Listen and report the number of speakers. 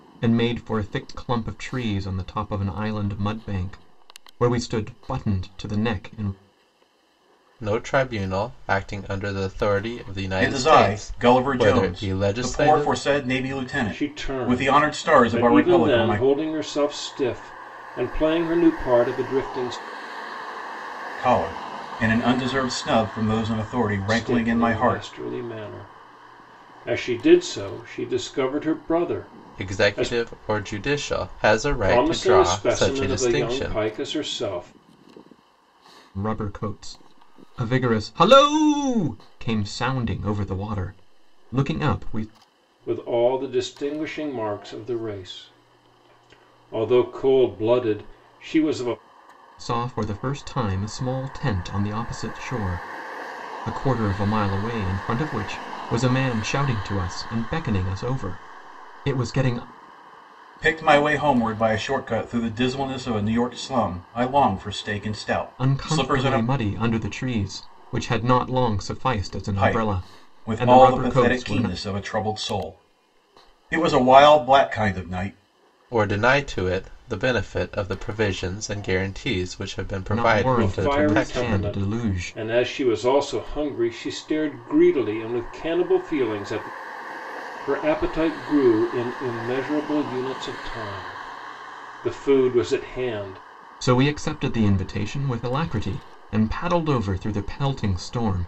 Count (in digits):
4